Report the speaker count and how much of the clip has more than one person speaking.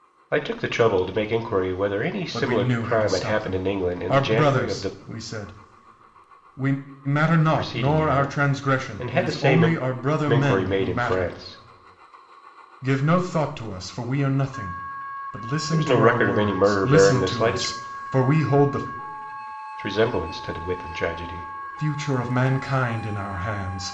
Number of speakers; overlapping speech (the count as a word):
two, about 34%